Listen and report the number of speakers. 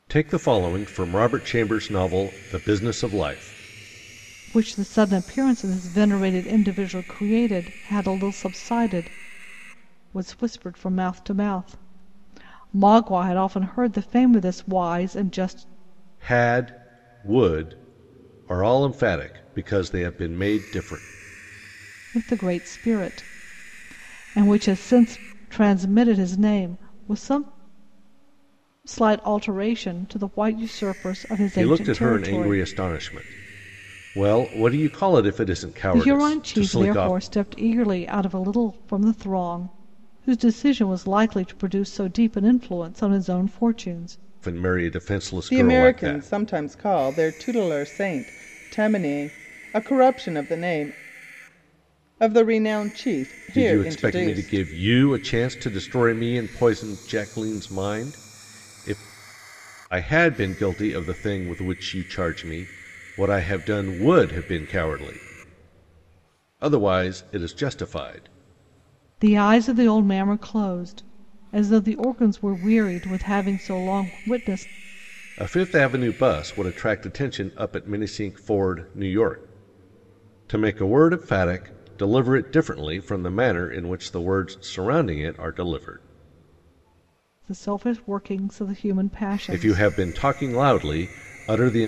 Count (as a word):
two